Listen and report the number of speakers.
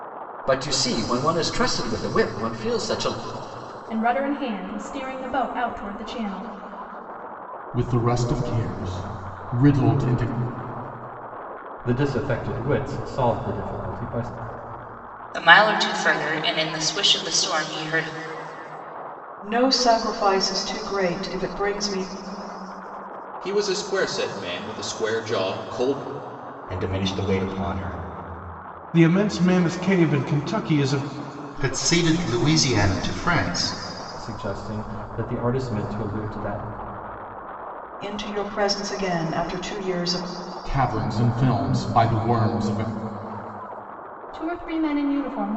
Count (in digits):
10